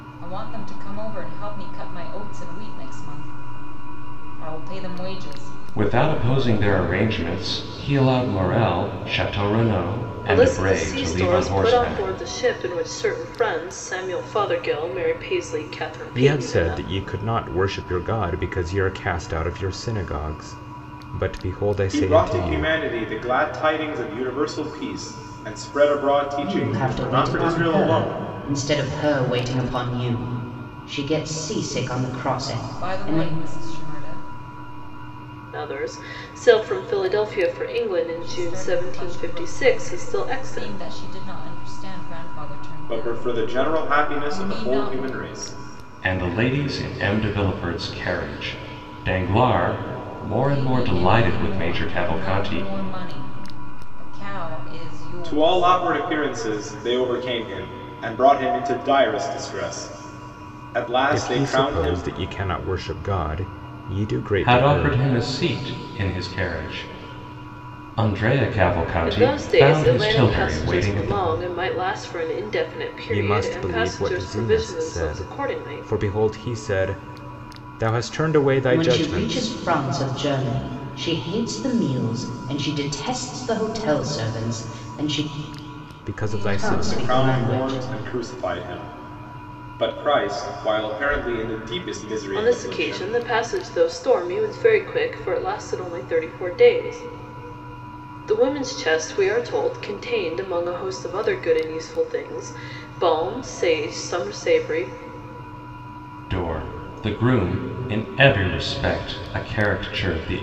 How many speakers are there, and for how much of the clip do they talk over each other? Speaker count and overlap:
6, about 22%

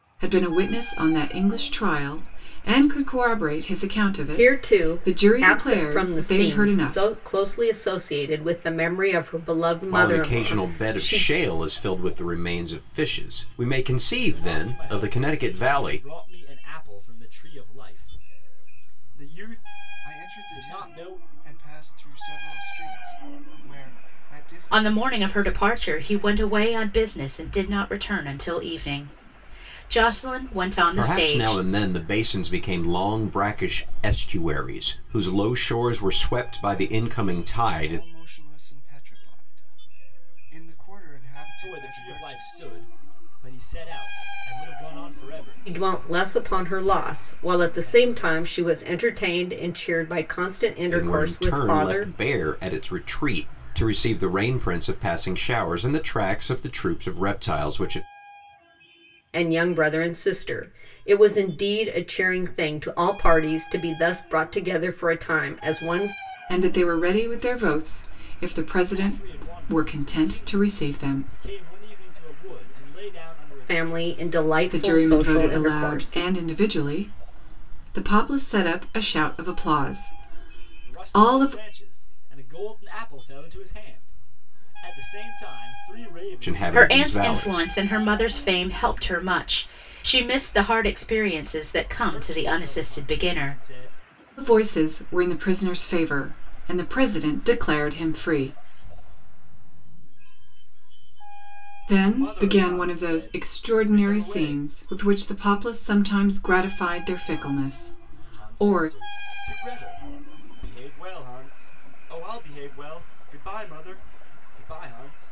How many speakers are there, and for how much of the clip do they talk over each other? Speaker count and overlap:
6, about 26%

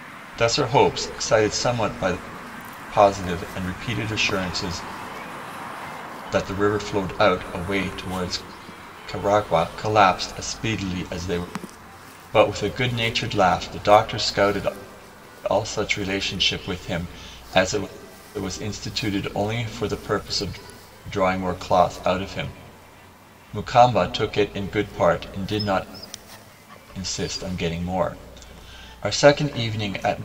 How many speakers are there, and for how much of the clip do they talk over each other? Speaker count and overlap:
1, no overlap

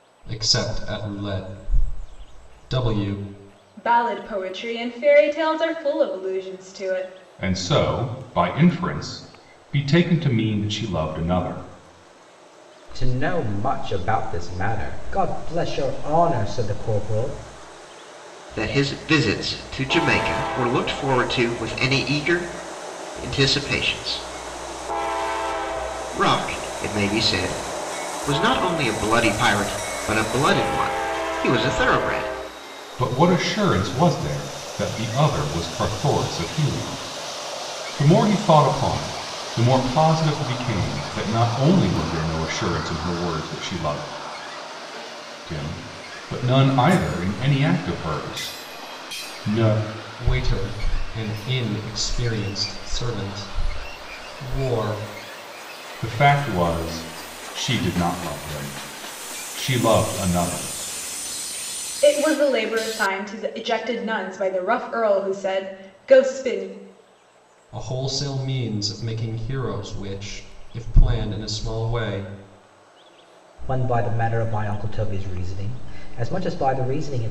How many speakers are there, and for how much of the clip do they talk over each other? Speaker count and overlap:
5, no overlap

